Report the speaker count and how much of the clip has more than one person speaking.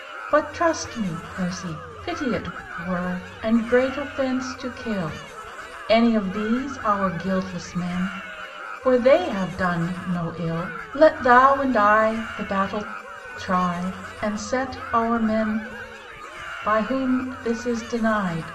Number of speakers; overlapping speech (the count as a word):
one, no overlap